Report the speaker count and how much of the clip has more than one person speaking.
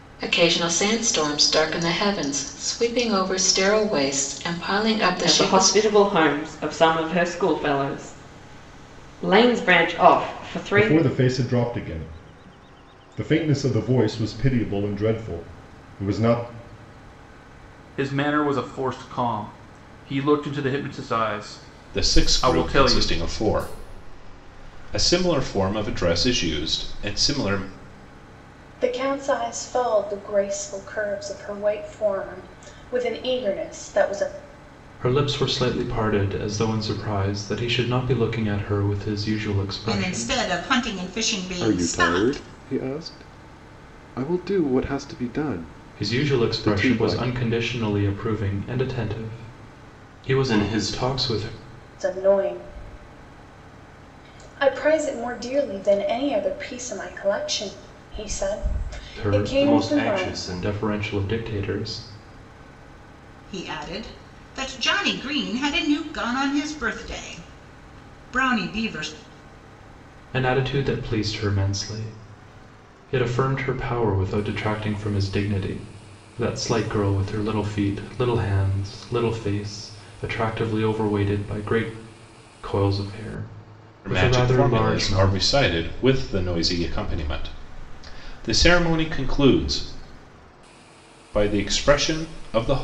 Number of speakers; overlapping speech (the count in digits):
9, about 8%